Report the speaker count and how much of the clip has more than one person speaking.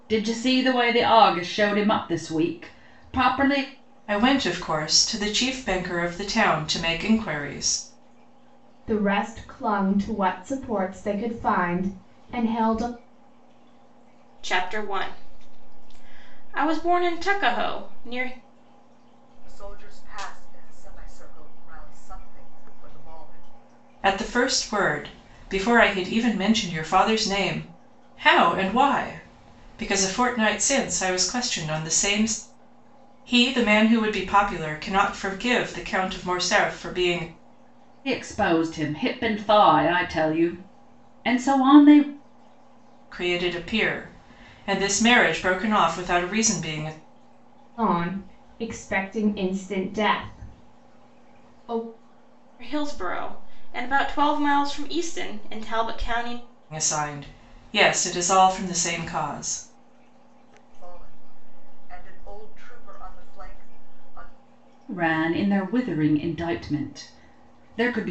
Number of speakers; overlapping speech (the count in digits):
5, no overlap